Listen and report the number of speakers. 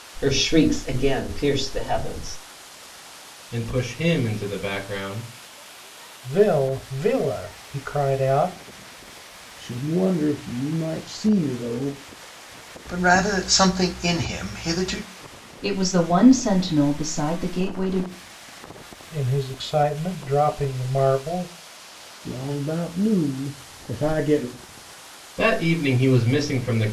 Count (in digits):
6